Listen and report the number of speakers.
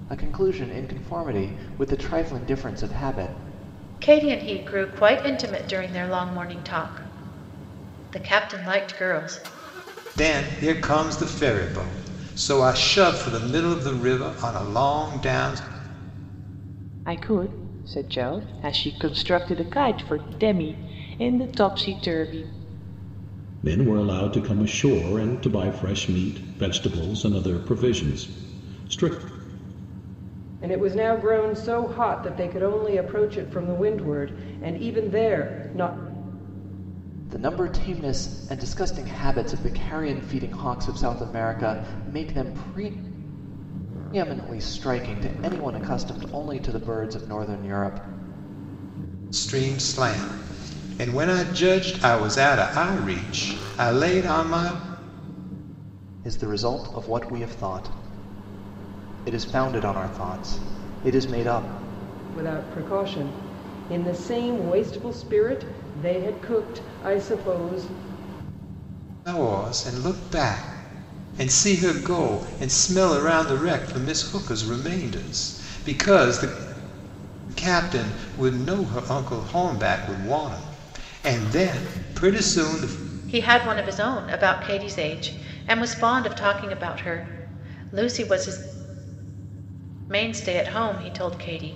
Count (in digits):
6